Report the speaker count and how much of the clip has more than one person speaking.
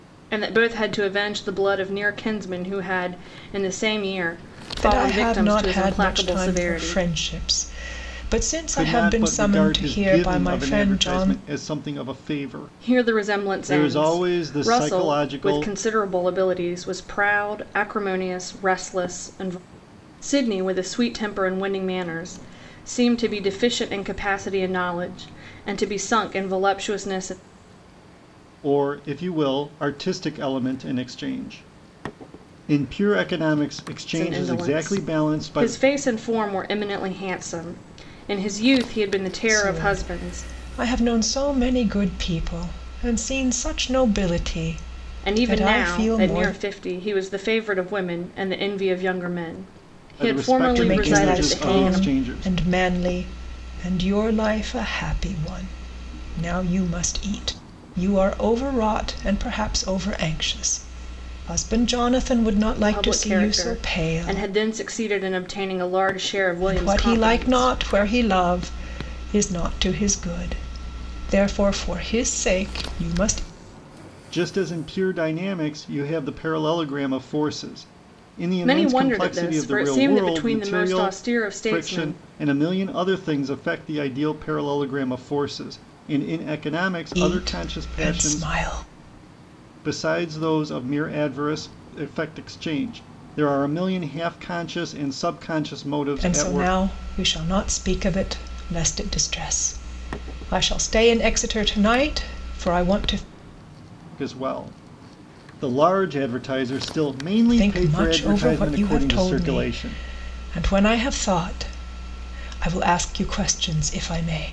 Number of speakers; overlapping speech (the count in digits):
3, about 22%